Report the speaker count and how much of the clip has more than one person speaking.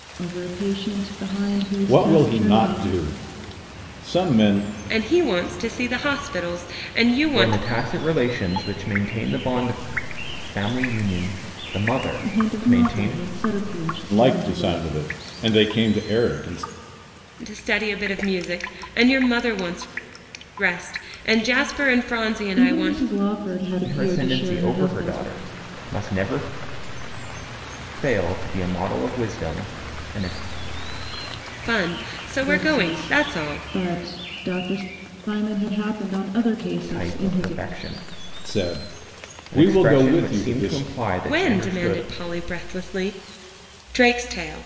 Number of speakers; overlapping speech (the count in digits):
4, about 21%